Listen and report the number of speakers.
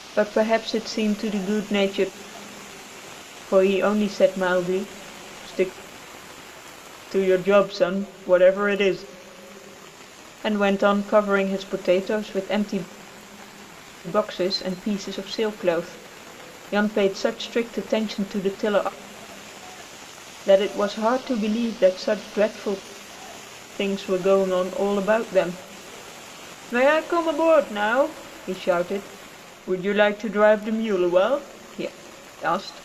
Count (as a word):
one